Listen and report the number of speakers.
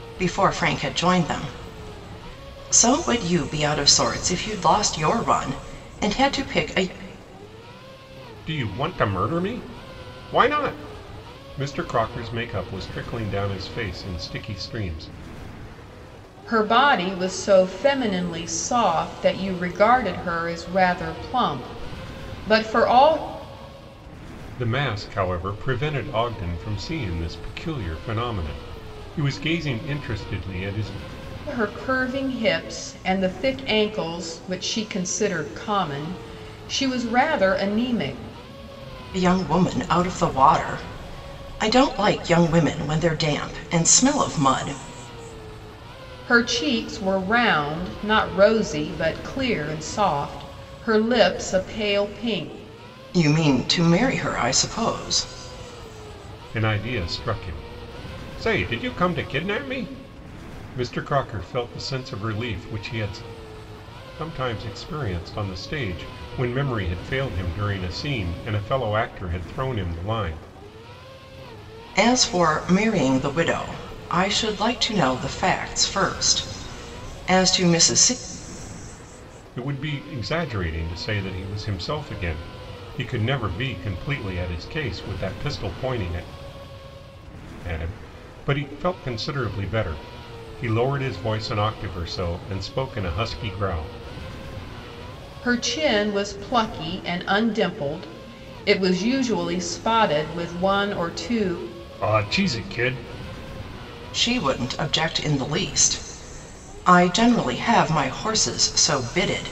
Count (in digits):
3